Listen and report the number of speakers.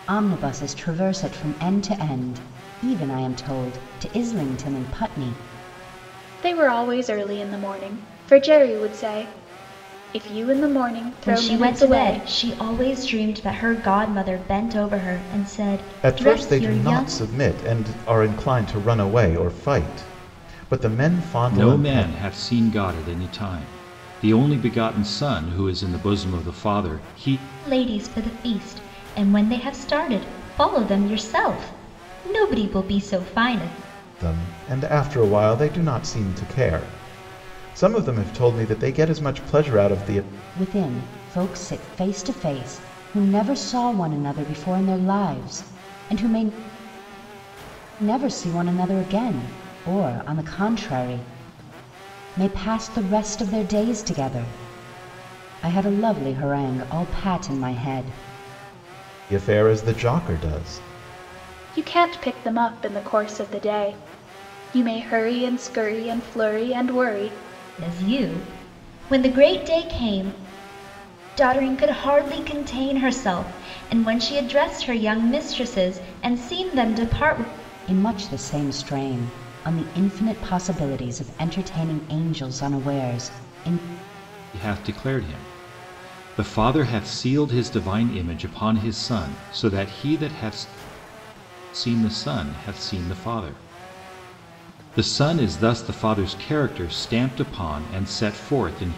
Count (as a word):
five